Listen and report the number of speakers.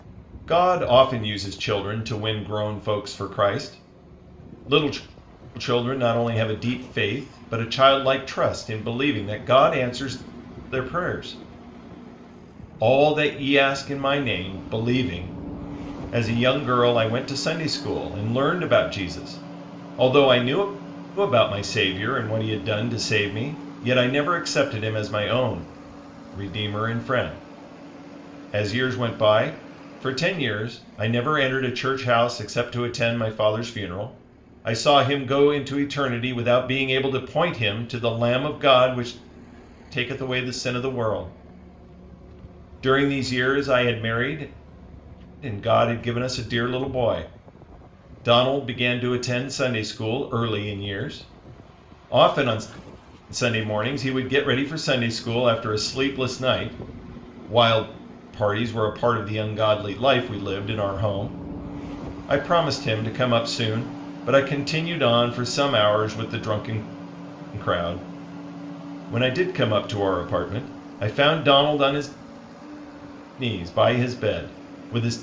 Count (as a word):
one